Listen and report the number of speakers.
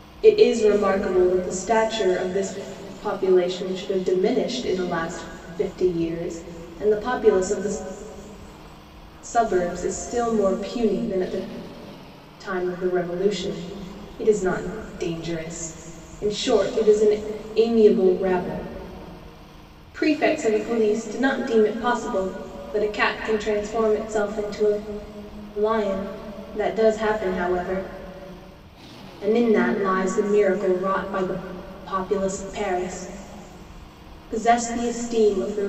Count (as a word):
one